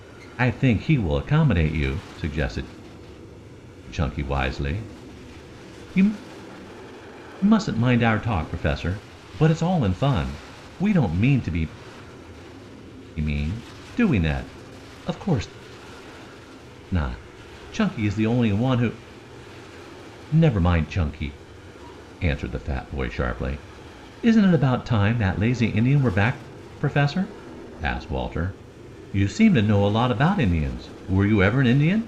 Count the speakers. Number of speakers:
one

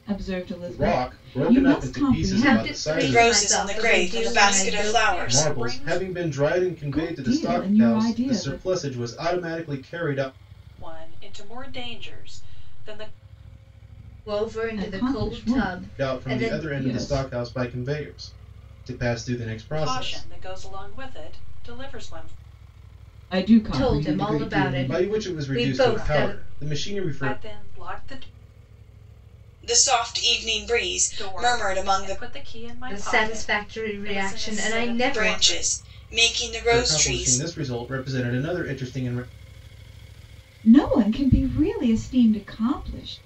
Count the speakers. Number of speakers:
five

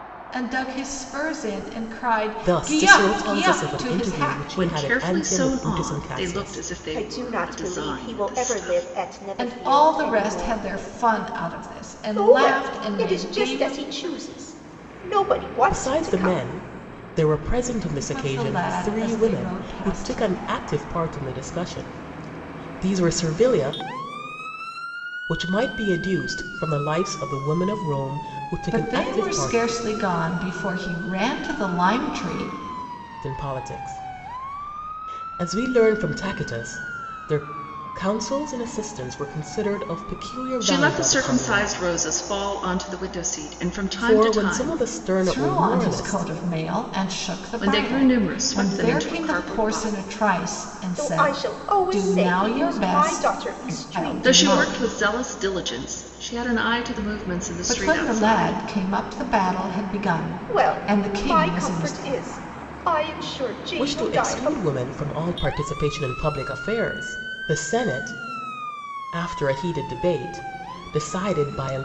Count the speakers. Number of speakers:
four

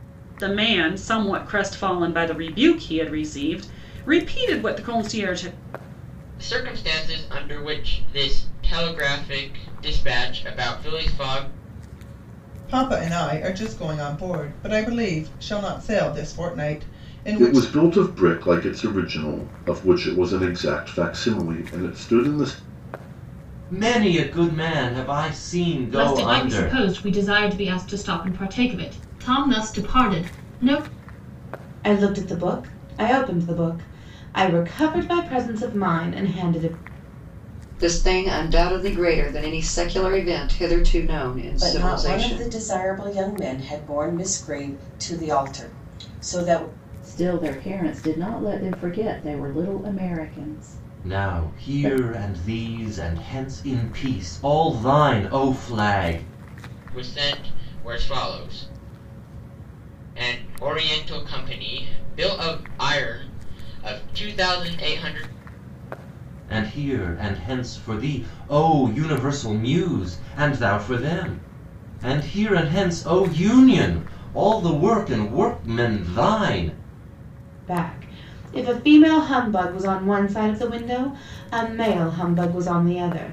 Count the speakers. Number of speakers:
ten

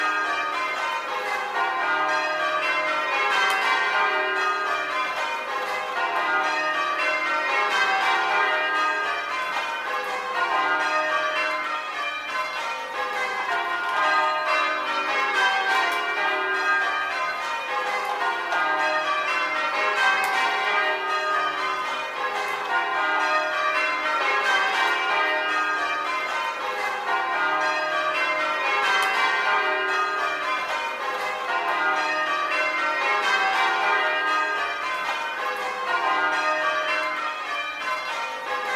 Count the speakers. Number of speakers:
zero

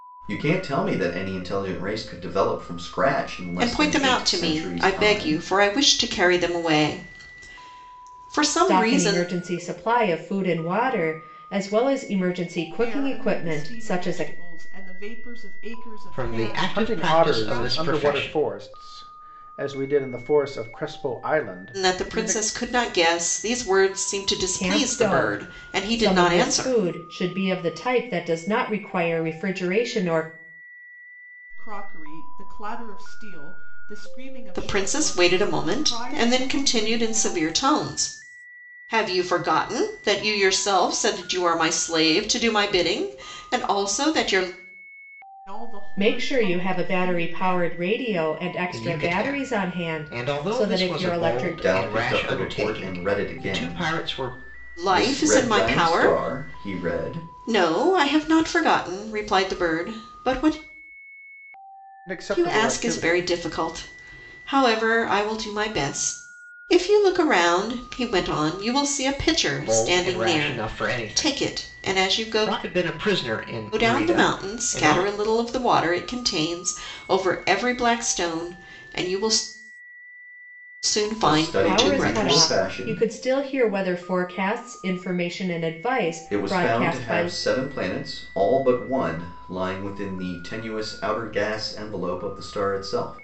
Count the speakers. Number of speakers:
six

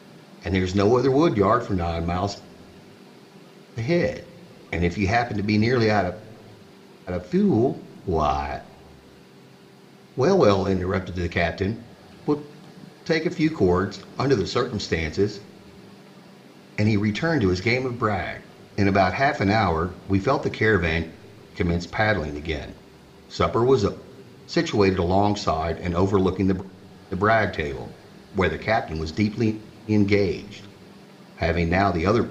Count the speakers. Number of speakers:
one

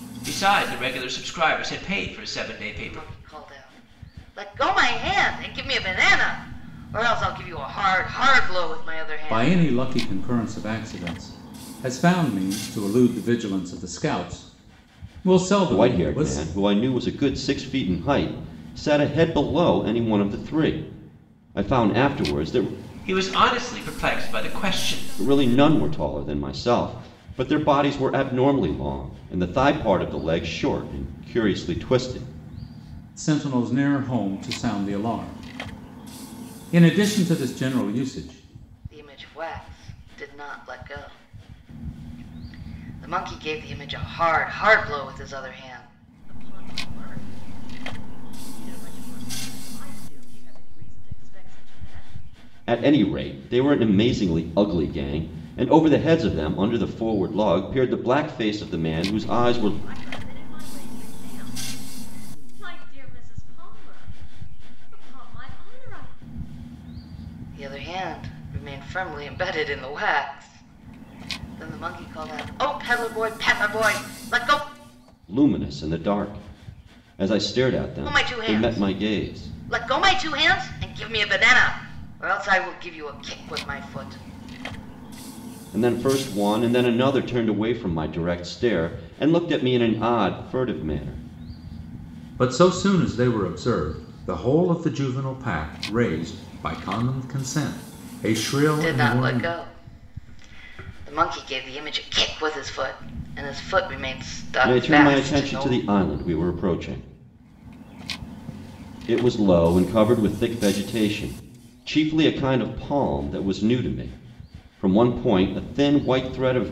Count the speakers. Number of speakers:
five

